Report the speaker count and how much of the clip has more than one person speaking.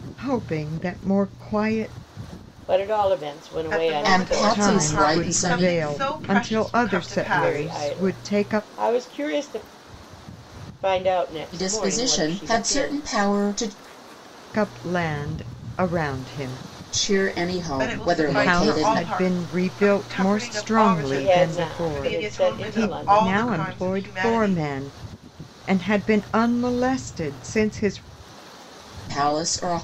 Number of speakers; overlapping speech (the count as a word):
four, about 44%